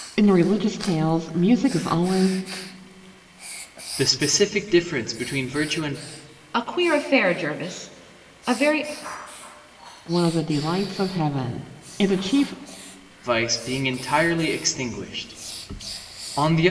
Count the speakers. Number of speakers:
3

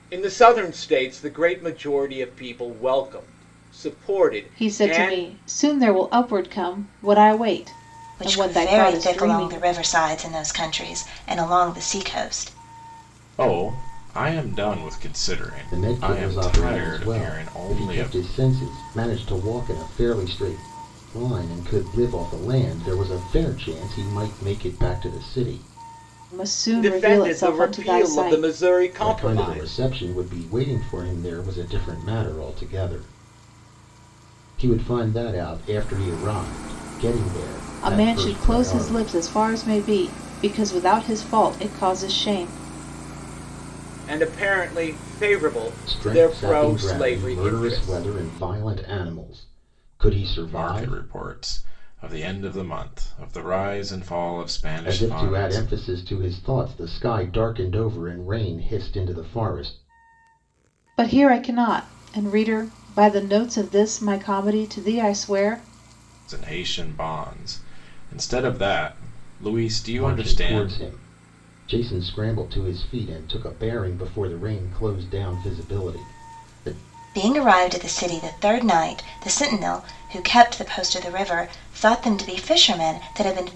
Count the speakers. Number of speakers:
5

